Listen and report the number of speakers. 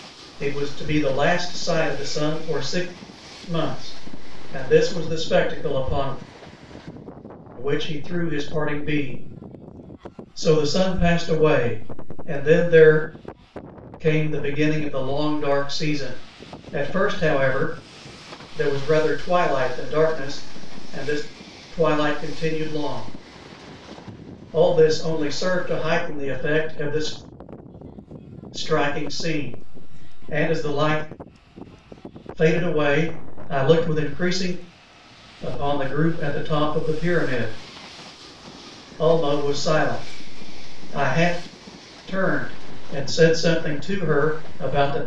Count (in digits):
1